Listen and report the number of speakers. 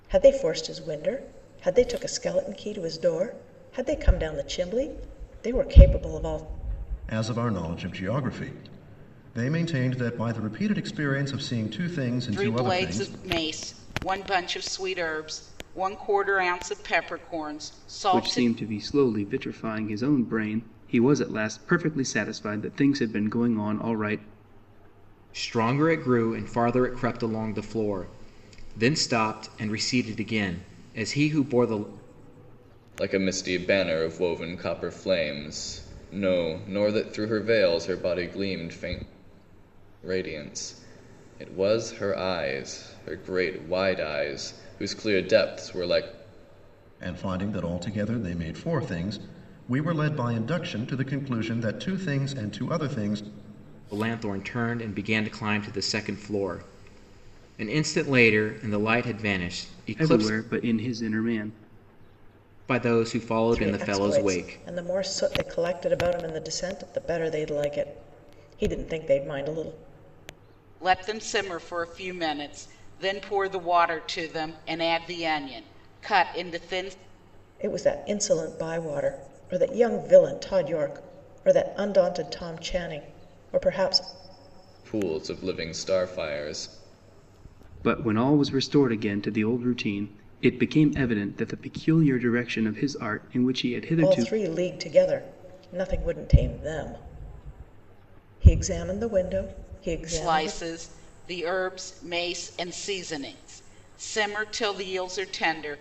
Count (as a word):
six